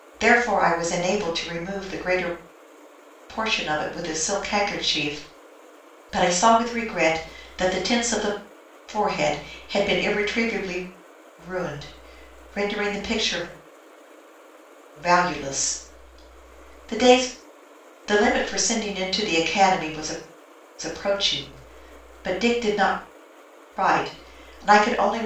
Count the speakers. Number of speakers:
one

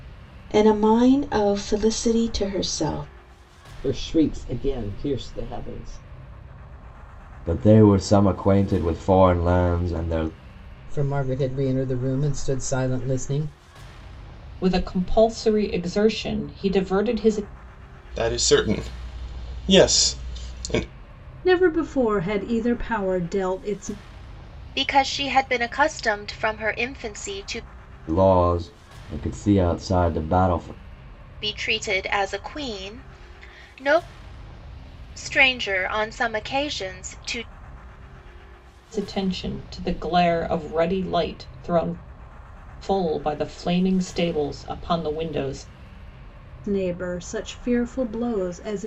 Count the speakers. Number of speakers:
eight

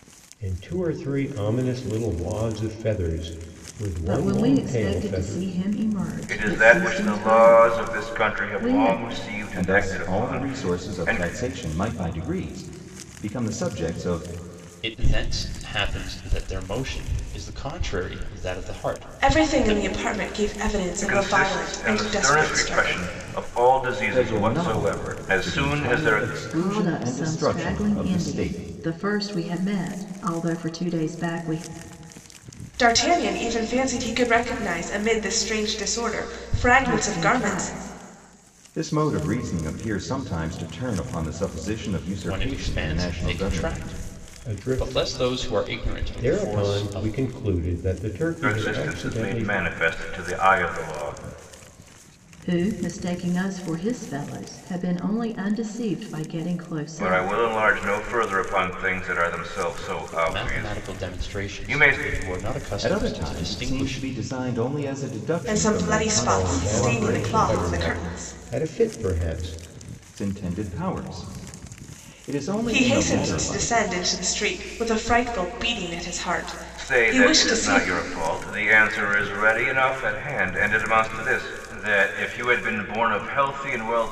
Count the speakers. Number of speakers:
six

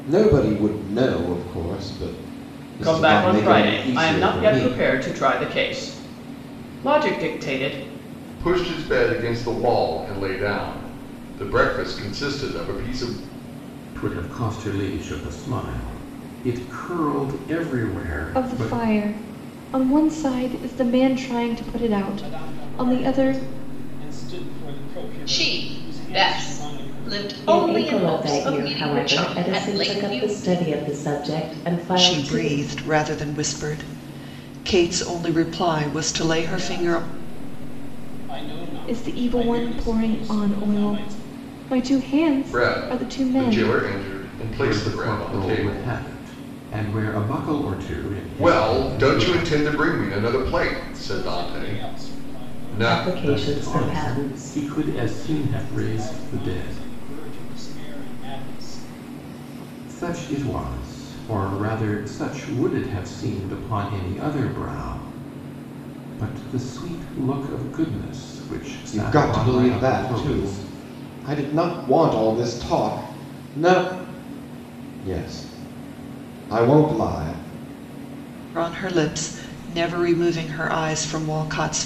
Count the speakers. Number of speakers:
nine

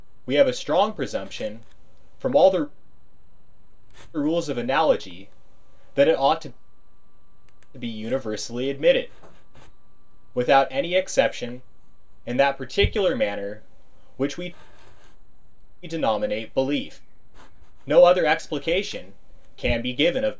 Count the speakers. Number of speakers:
one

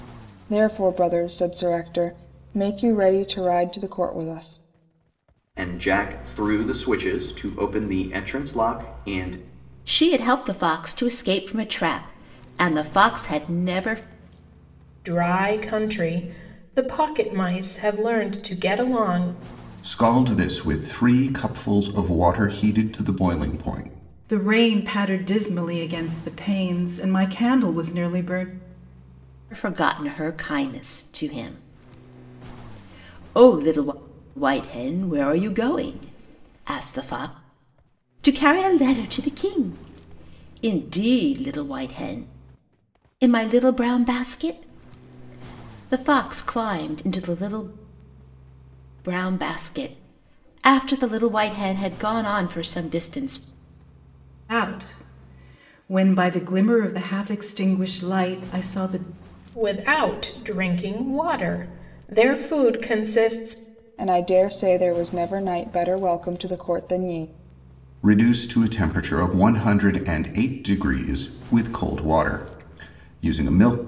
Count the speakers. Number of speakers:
six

